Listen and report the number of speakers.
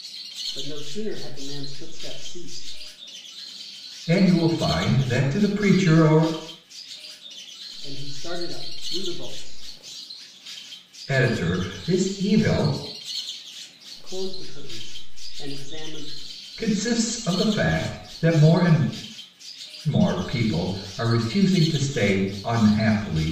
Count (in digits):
2